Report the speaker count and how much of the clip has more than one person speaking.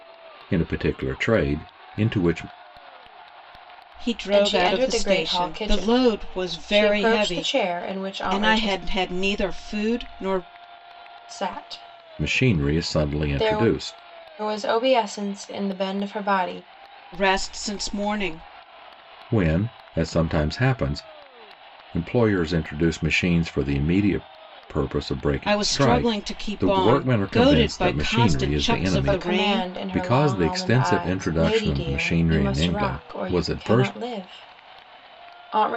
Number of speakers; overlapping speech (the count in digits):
3, about 36%